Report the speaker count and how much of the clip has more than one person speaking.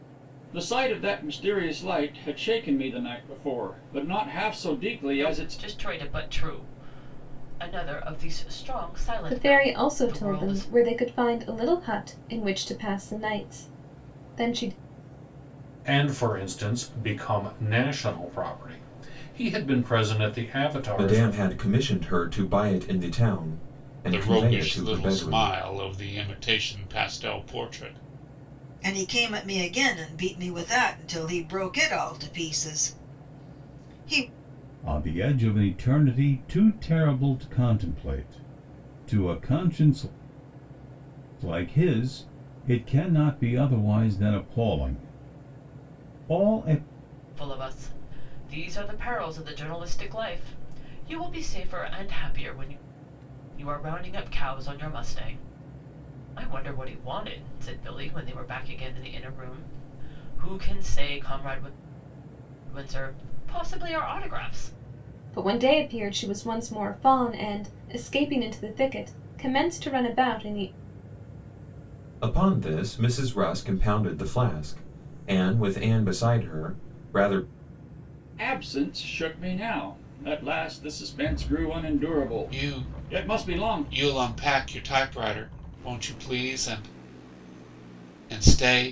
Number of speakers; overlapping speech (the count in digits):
8, about 6%